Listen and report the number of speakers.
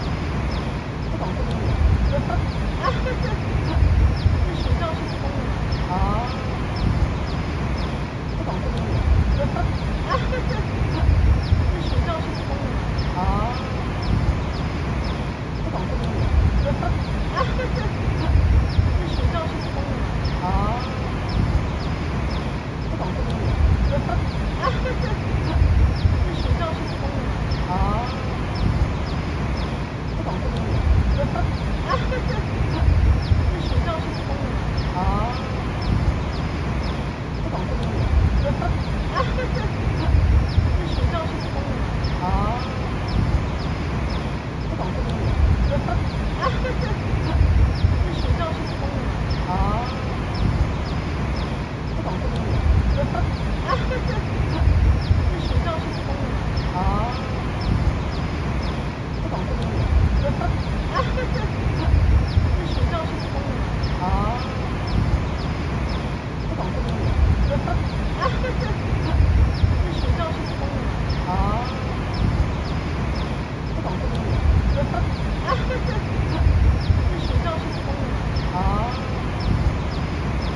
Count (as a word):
zero